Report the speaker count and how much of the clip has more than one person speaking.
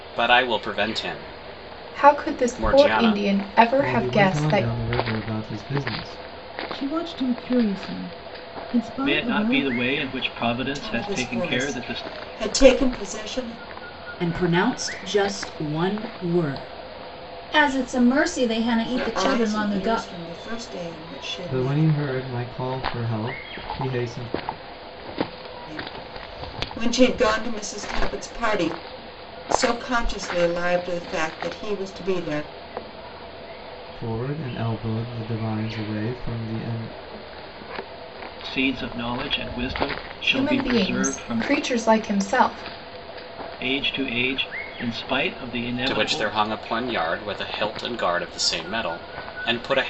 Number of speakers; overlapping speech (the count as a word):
eight, about 16%